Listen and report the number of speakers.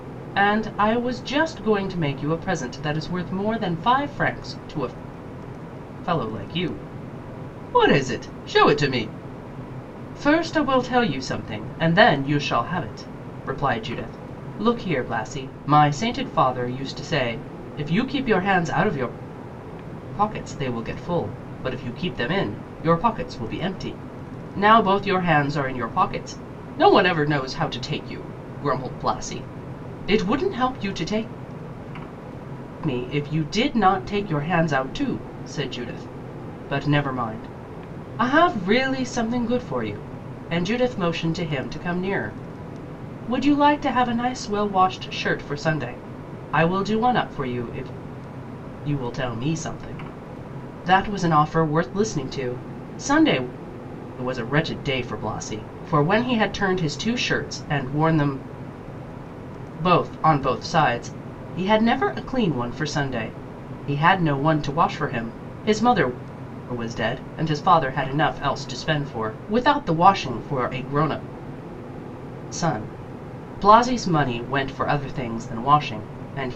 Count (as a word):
one